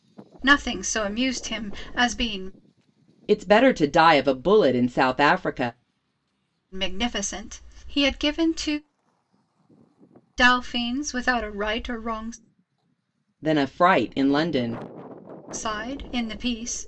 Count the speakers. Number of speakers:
two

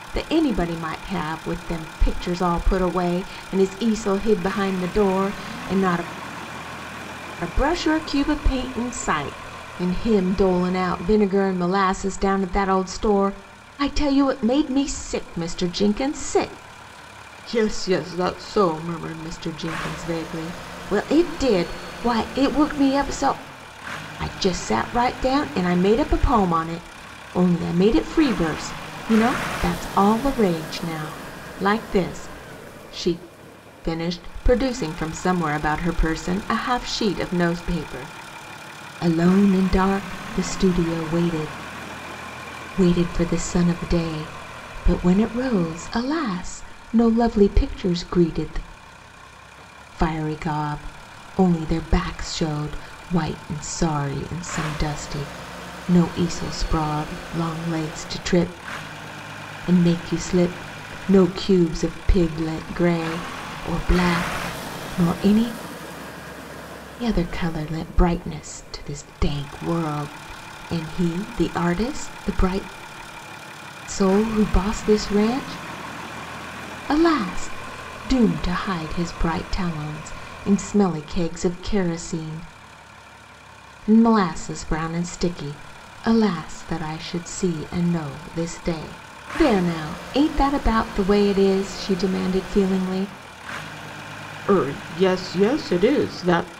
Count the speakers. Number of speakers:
one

